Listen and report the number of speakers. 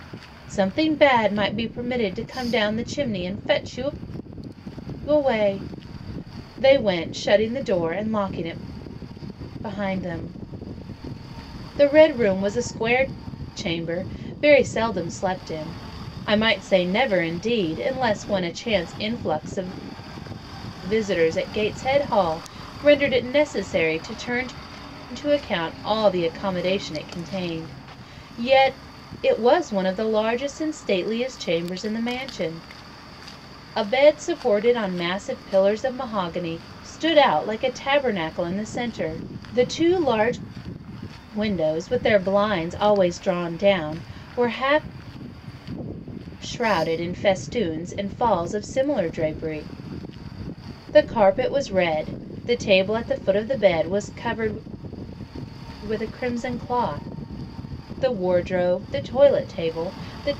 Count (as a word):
one